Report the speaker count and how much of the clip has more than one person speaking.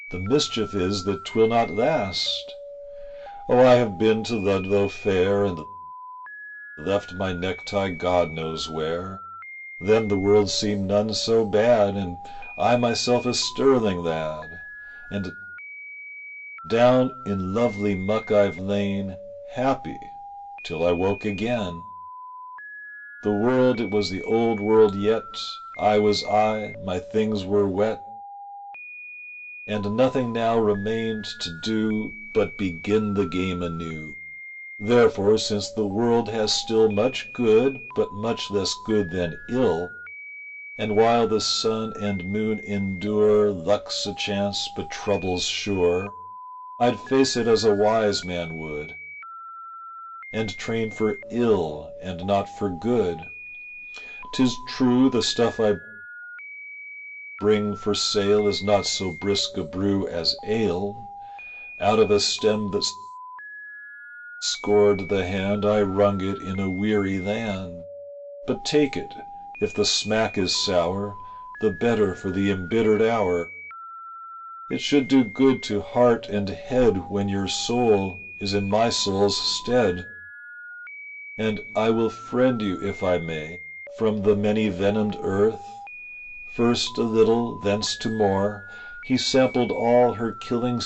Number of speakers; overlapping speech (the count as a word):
one, no overlap